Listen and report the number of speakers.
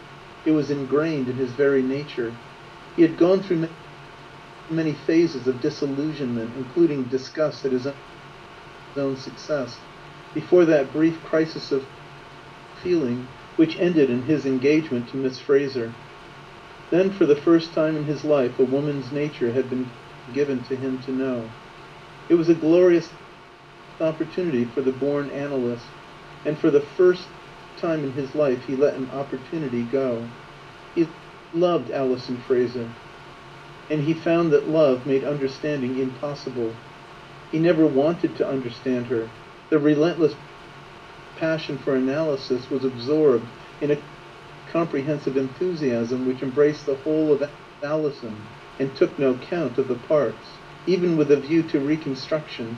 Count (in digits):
1